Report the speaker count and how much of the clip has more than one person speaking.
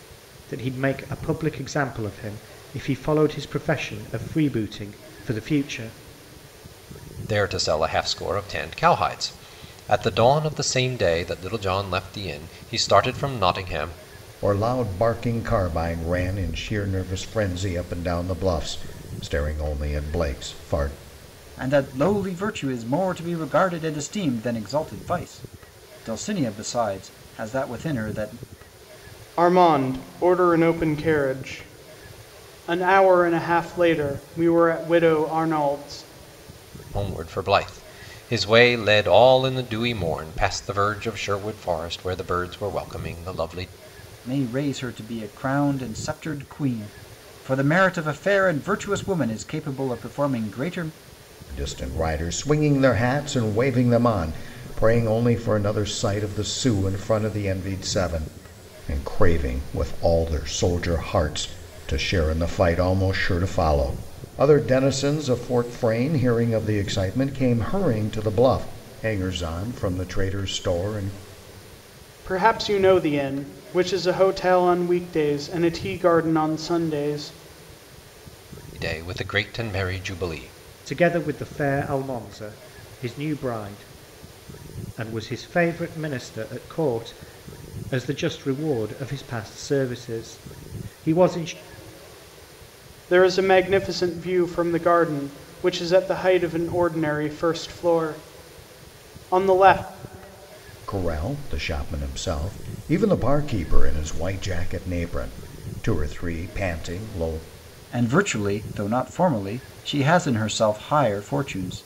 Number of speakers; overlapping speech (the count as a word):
five, no overlap